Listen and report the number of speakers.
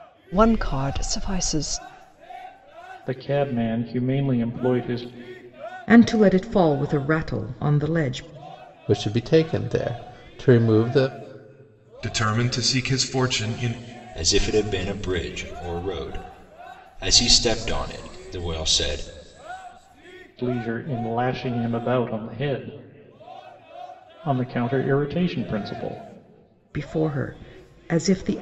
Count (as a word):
six